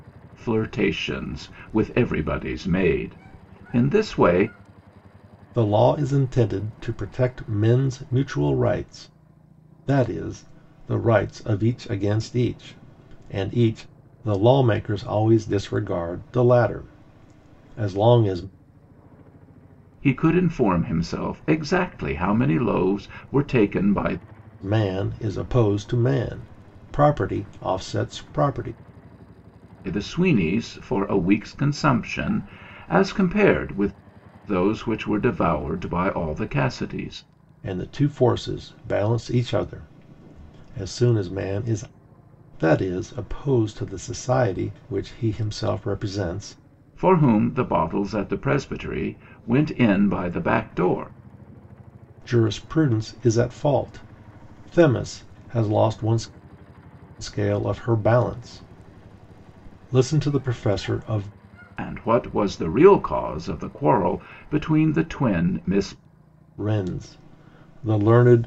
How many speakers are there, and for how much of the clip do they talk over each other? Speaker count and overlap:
two, no overlap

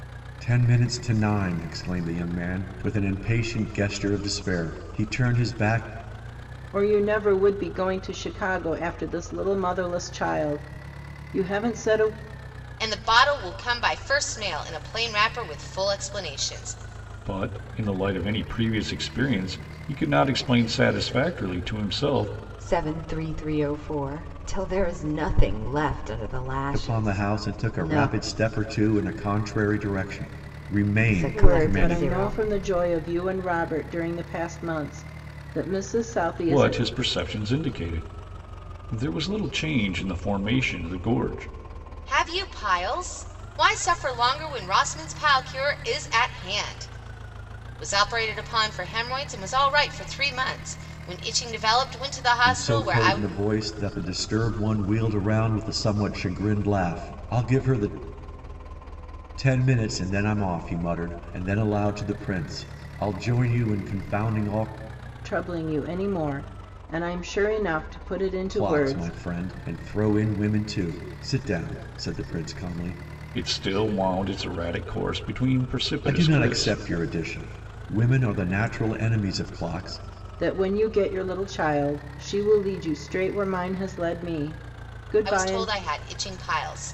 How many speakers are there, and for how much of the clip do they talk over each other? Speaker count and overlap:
five, about 7%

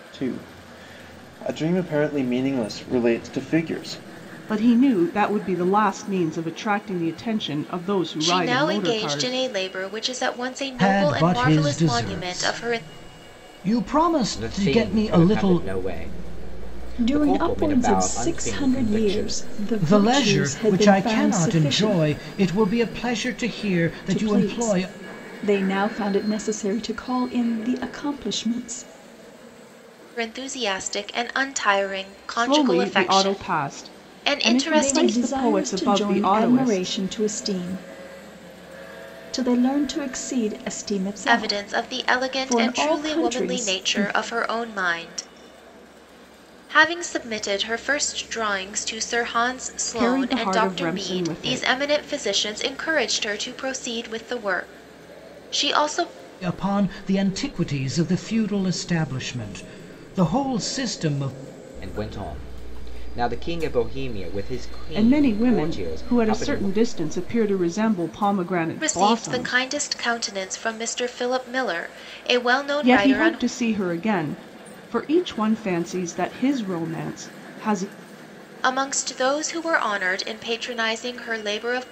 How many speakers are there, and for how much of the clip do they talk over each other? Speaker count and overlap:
six, about 28%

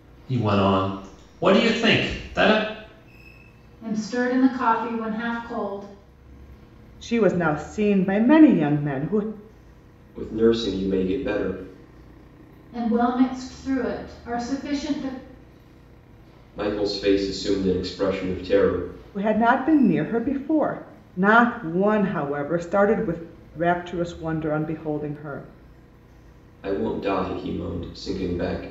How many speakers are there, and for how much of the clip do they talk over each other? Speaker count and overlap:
four, no overlap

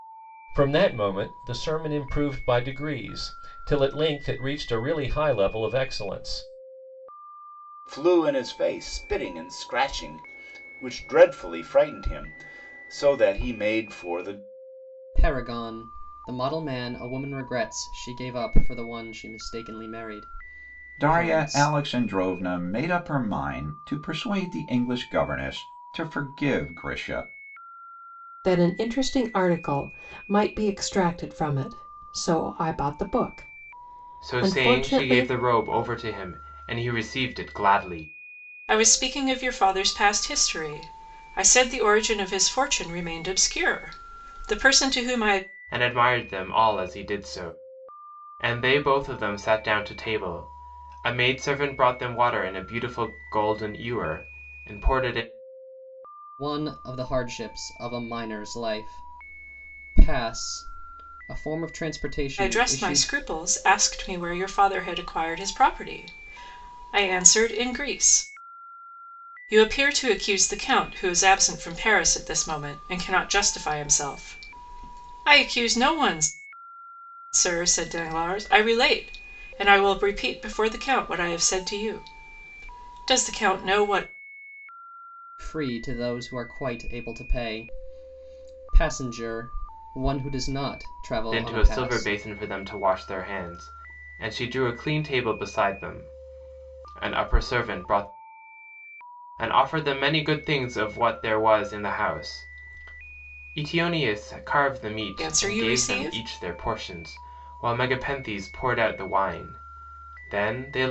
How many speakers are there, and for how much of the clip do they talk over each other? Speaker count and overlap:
seven, about 4%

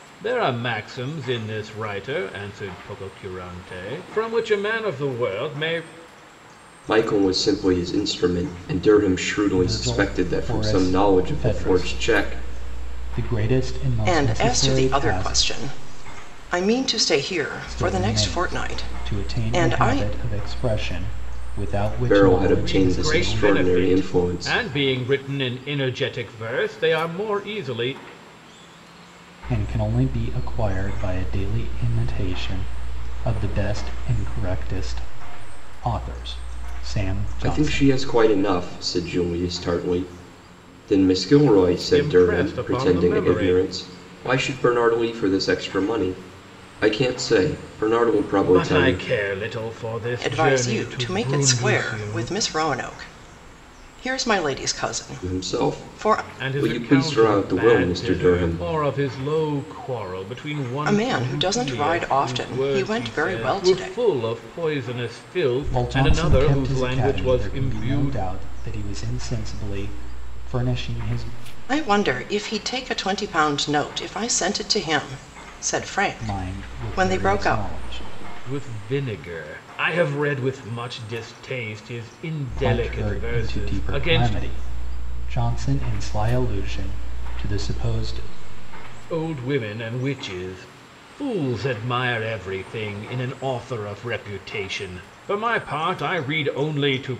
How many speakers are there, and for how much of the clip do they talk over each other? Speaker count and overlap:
four, about 27%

